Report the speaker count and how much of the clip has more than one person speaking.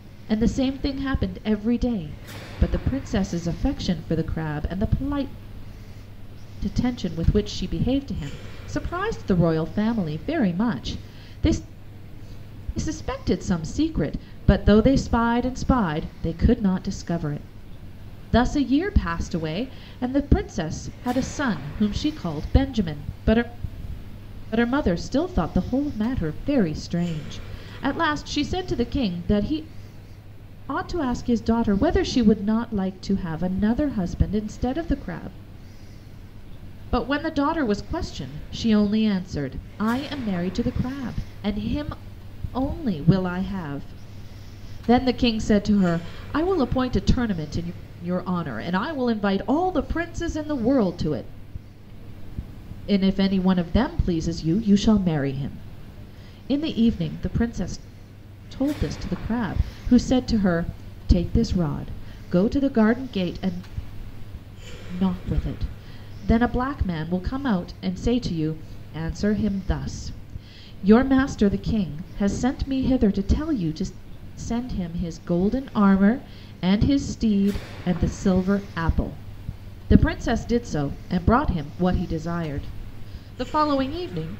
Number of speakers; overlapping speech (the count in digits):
1, no overlap